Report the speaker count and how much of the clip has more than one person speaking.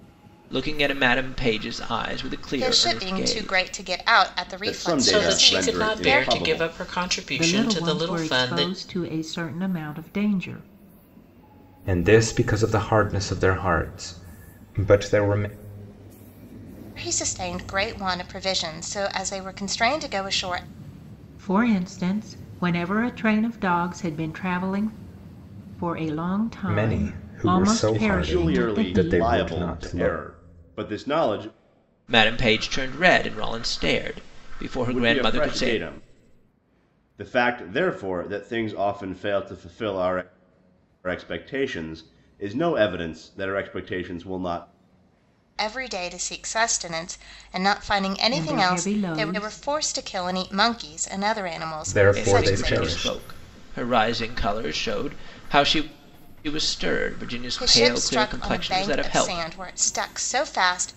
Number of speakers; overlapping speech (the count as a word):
six, about 23%